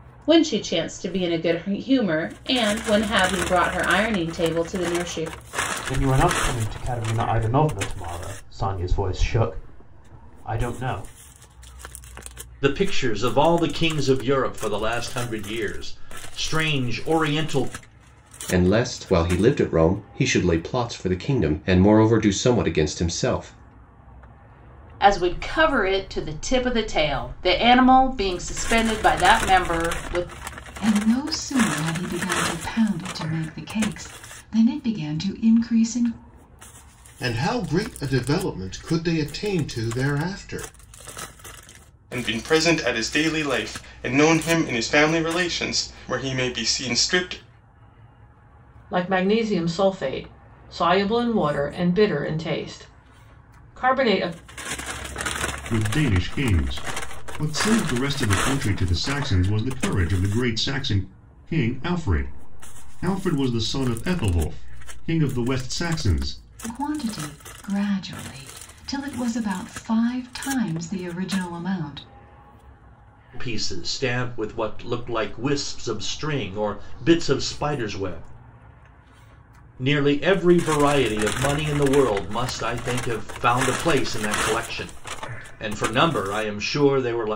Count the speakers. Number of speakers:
ten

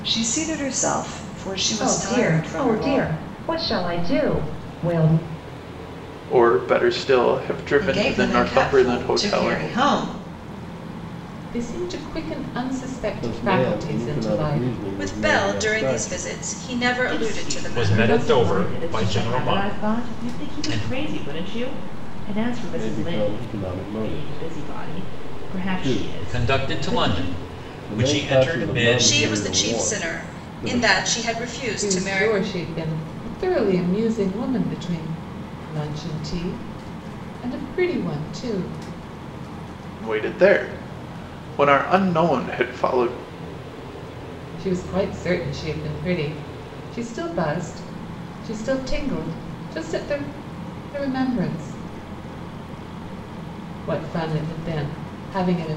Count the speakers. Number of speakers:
nine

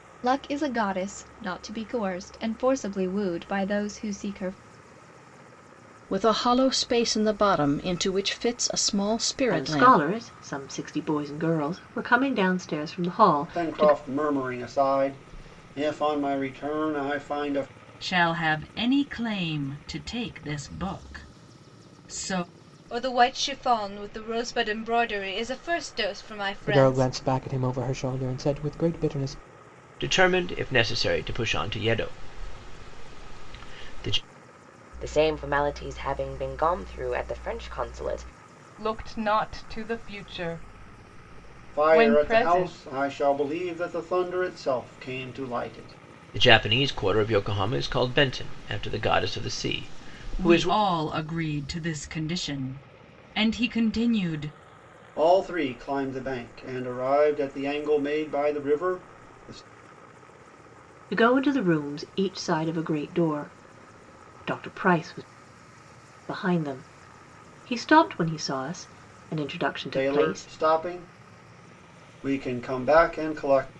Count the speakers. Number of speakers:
ten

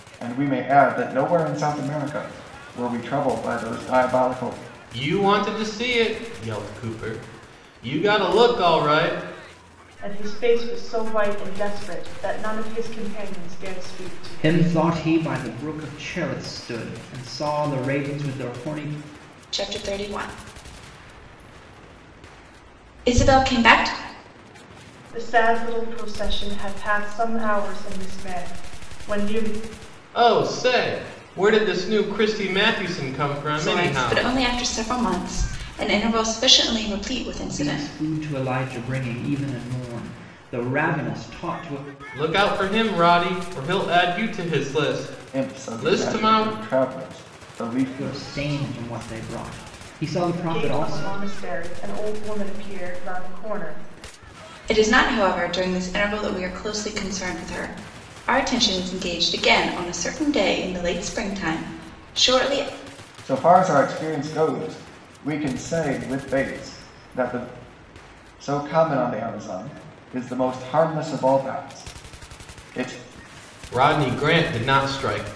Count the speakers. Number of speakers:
five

